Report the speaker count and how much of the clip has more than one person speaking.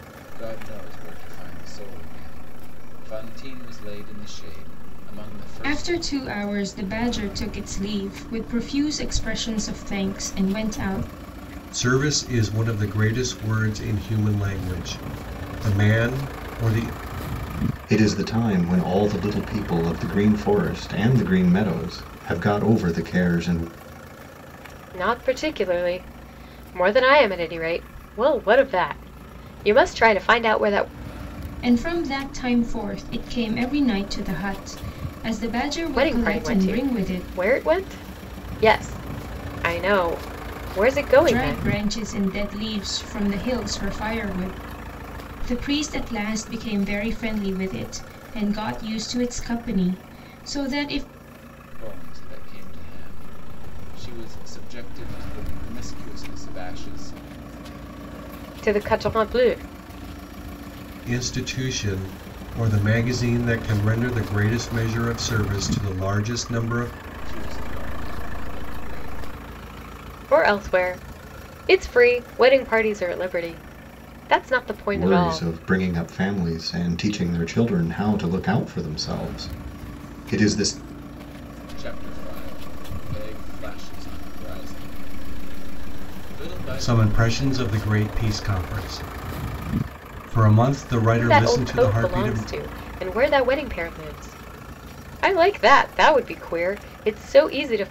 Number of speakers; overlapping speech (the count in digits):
5, about 5%